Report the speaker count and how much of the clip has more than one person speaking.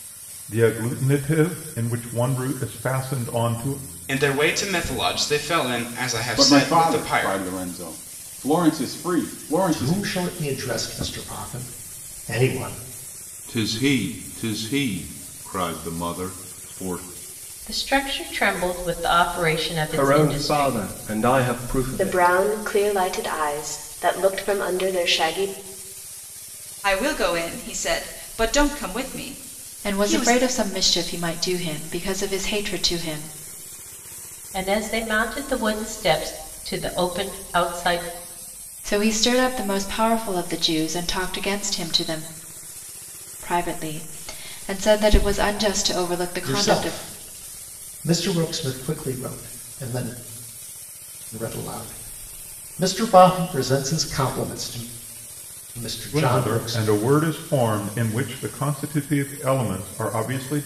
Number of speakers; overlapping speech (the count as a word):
ten, about 8%